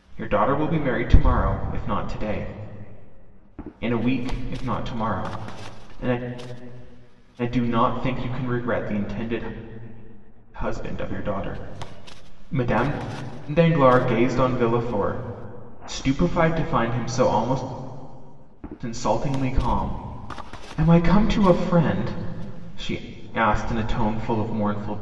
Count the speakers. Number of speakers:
1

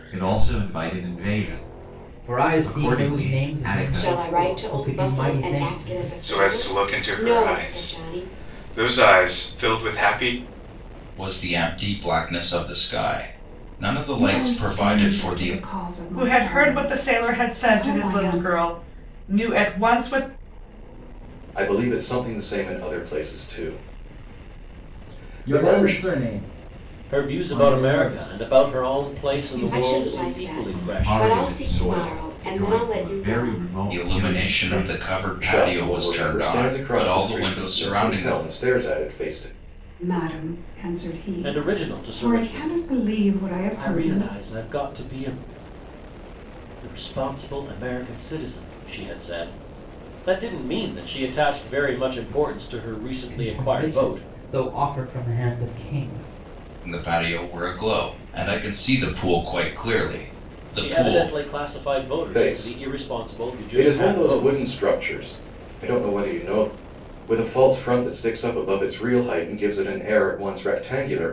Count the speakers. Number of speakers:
10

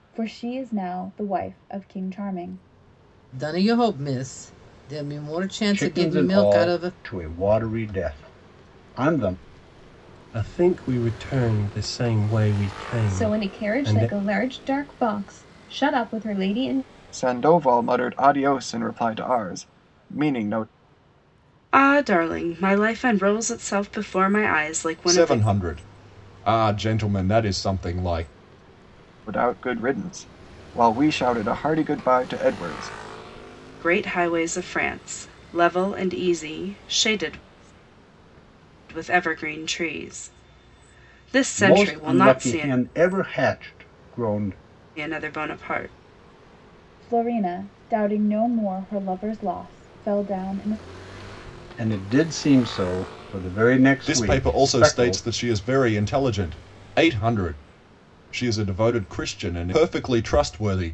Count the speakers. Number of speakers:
8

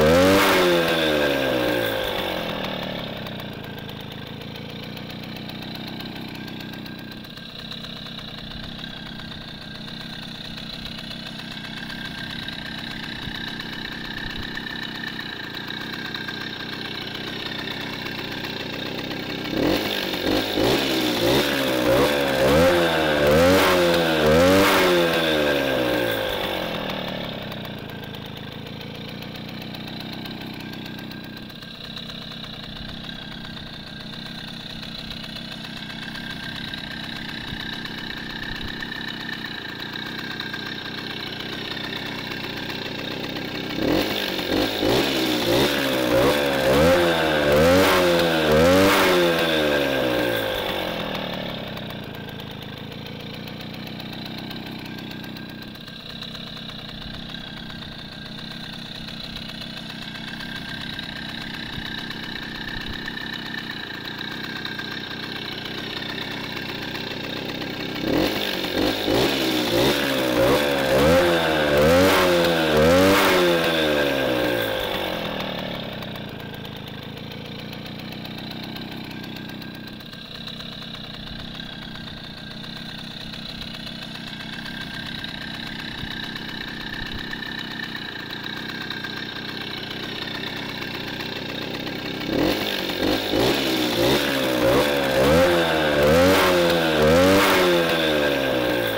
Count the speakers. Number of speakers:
0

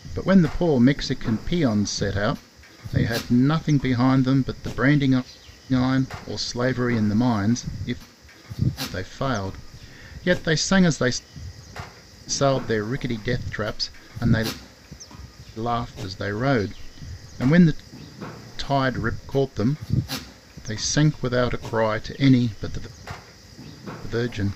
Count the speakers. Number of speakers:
1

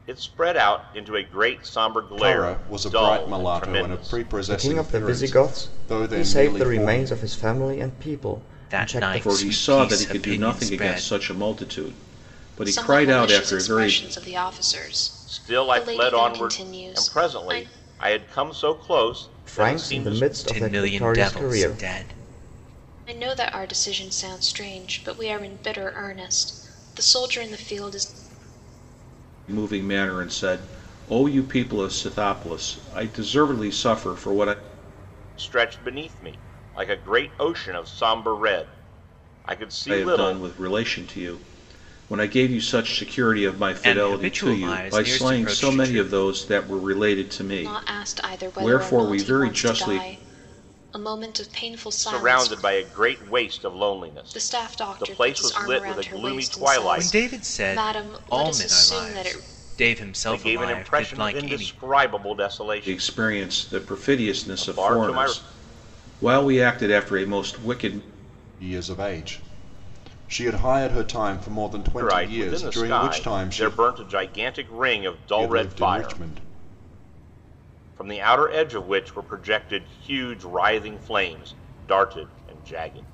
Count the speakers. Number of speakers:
6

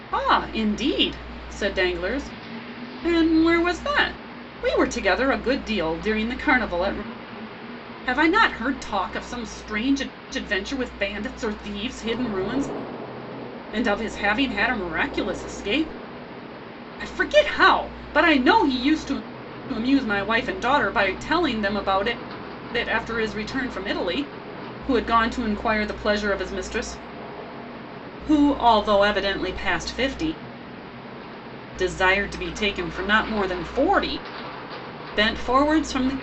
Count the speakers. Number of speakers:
1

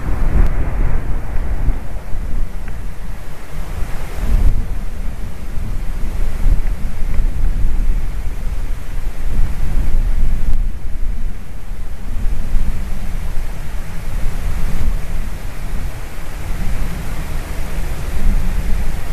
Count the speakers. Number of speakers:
0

